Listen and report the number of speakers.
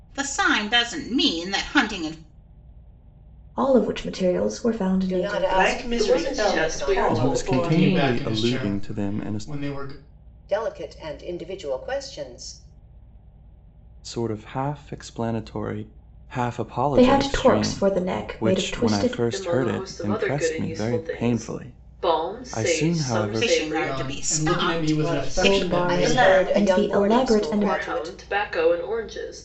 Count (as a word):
seven